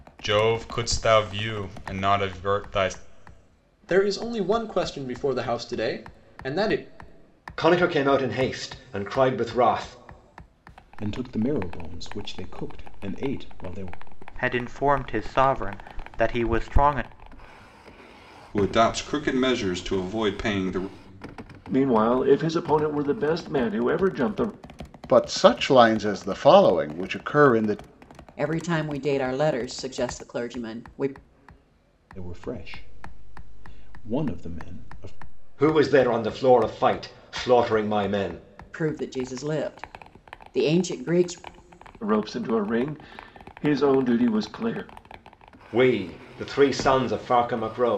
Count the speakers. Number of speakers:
nine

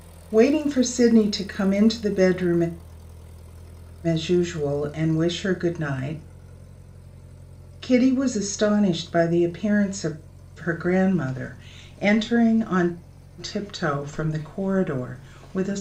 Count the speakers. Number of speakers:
one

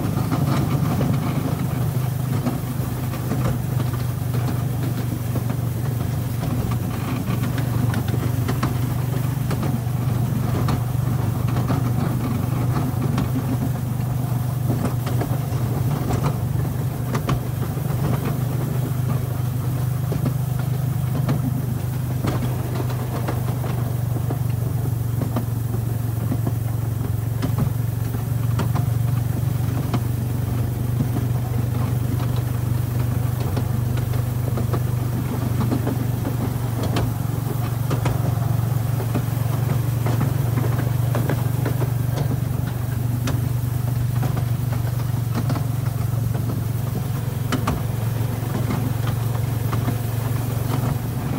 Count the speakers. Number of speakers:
zero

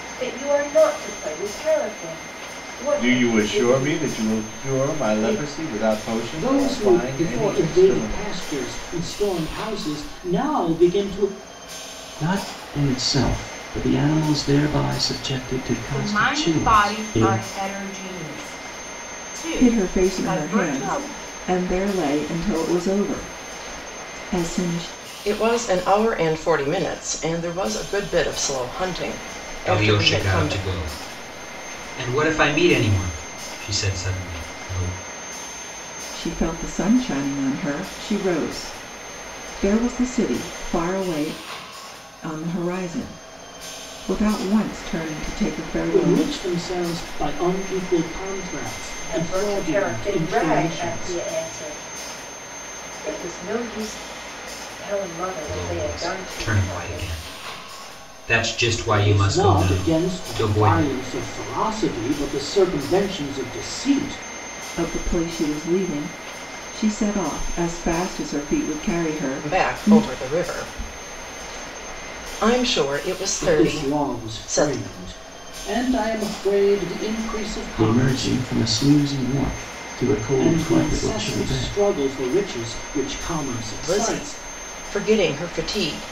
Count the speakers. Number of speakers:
eight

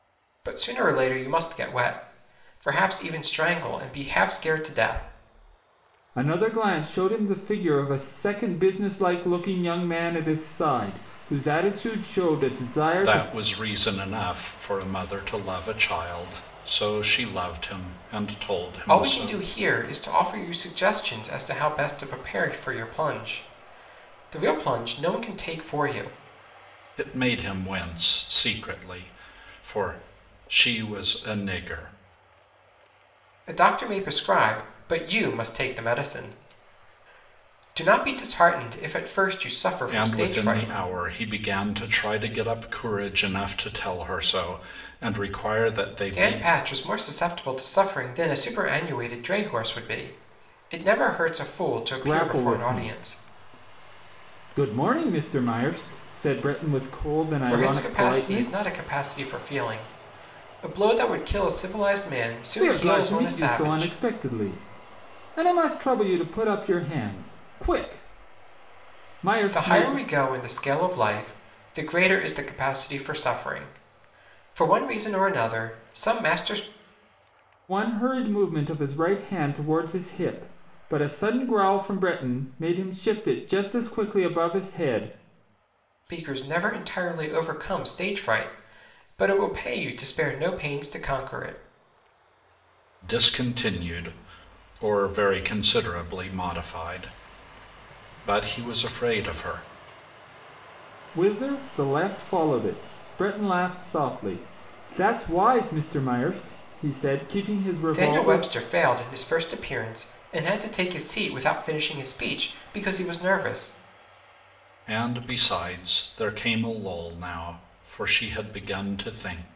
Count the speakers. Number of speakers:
three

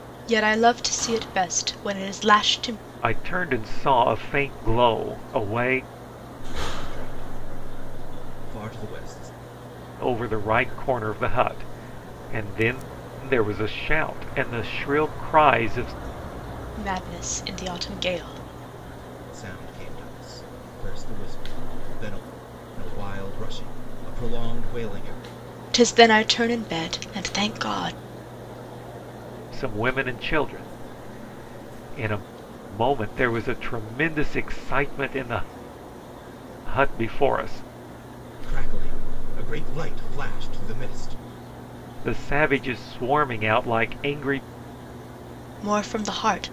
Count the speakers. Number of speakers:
three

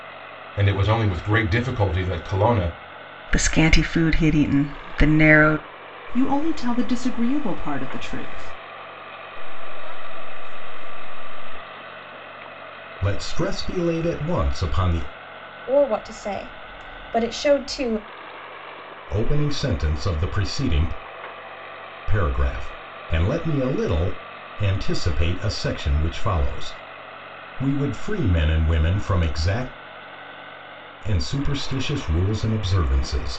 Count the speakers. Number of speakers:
six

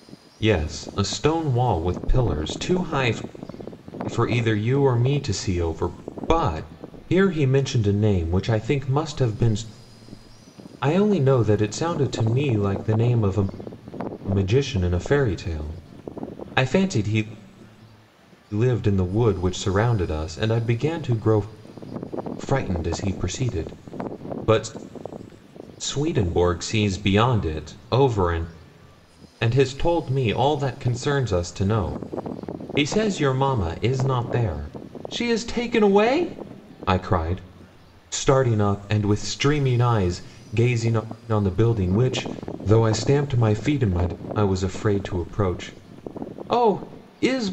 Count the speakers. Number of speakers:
one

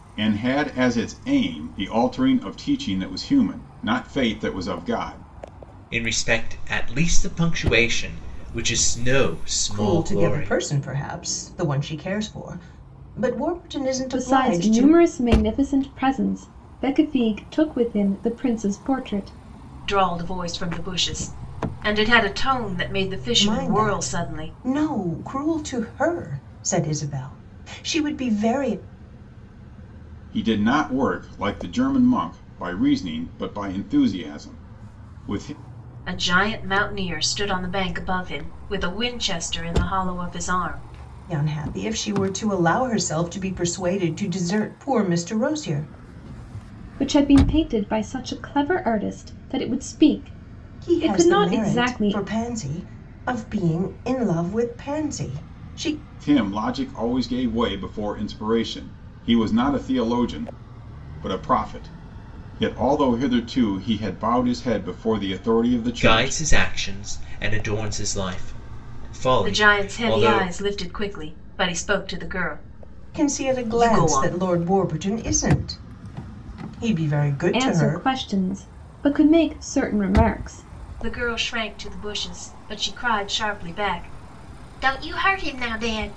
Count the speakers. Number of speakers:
five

